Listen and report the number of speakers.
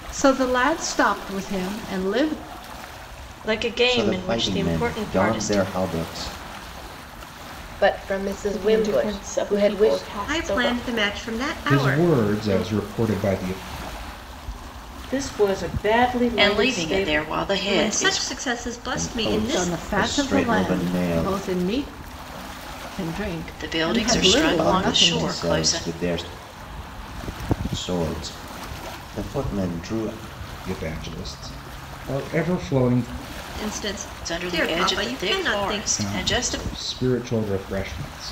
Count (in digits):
9